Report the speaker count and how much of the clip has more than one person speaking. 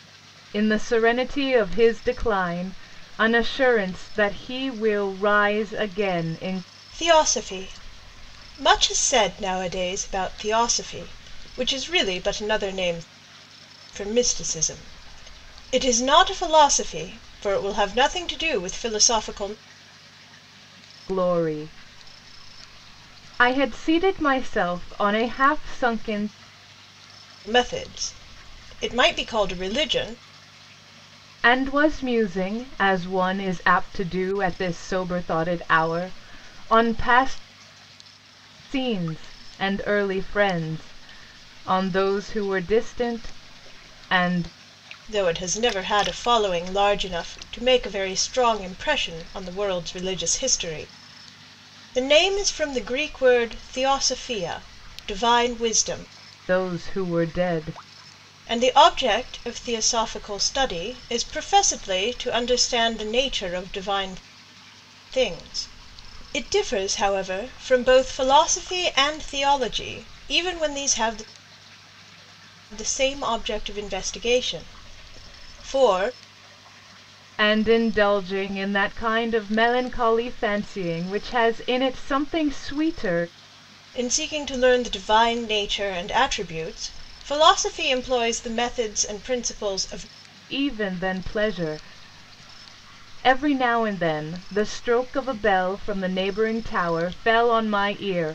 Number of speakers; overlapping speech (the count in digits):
2, no overlap